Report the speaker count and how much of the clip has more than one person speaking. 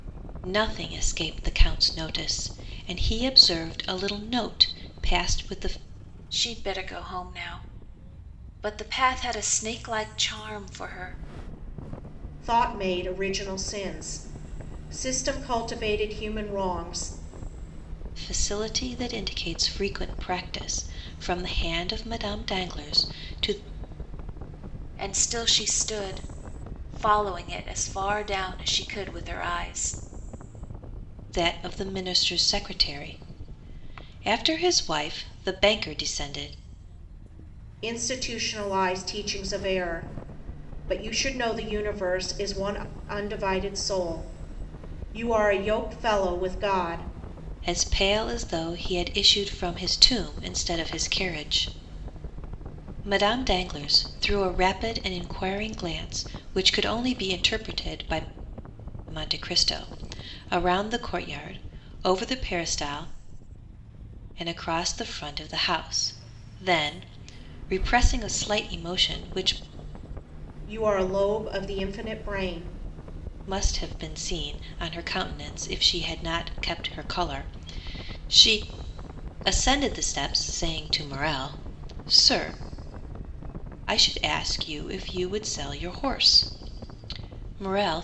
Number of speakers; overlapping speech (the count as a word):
three, no overlap